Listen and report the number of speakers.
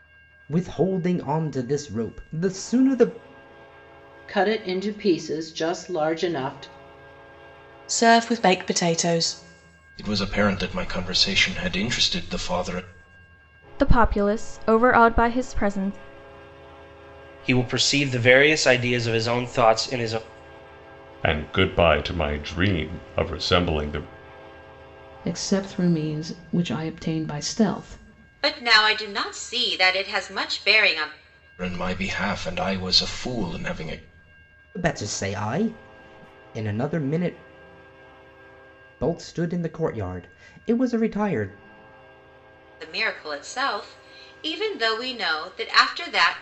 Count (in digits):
9